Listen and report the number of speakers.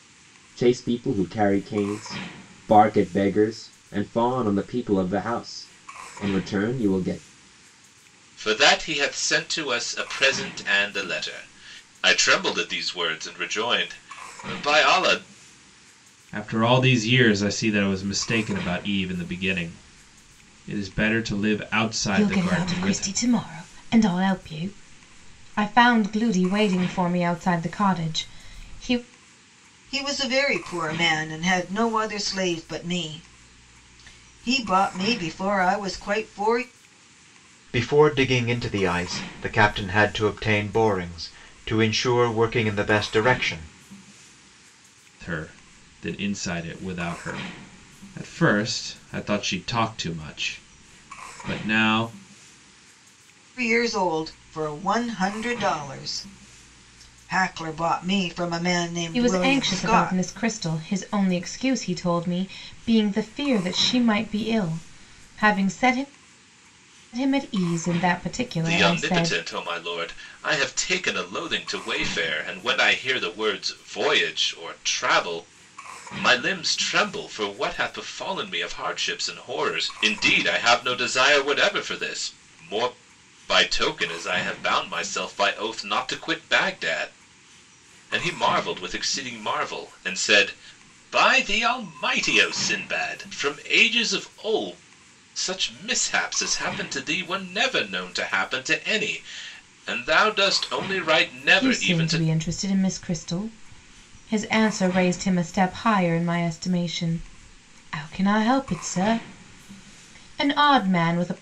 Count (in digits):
6